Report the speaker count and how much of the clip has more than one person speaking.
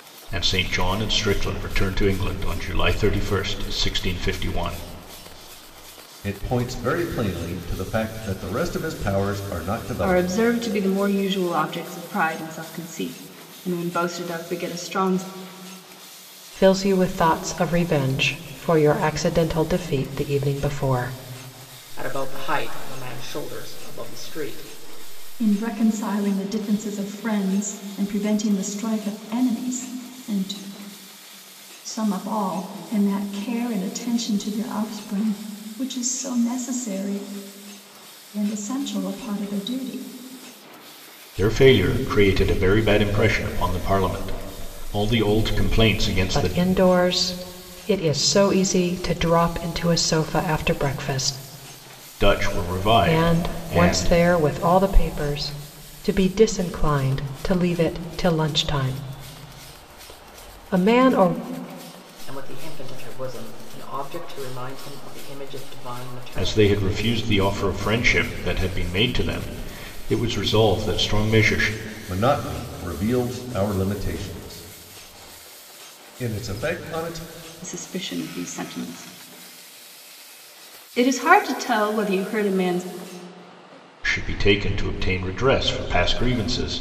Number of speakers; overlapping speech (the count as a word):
six, about 3%